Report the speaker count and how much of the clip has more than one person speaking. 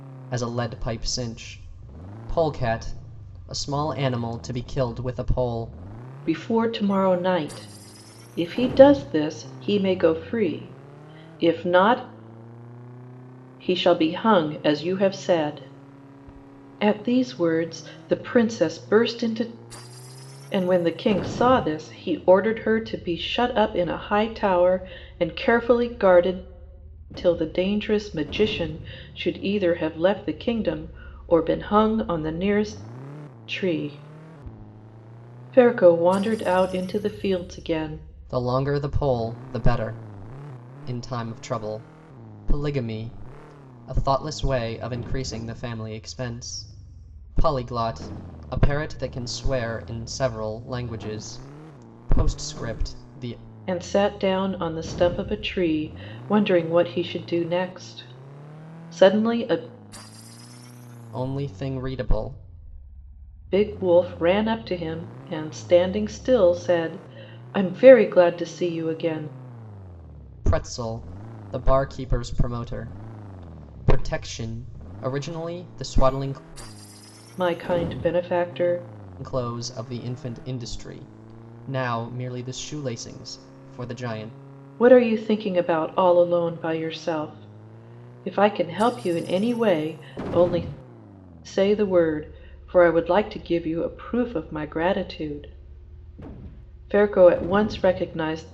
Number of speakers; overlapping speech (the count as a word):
two, no overlap